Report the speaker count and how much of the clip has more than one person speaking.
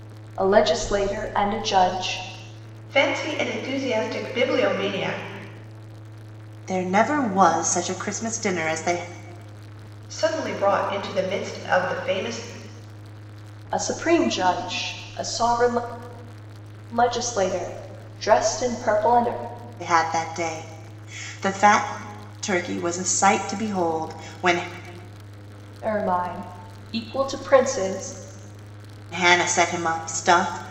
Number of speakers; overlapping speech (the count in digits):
3, no overlap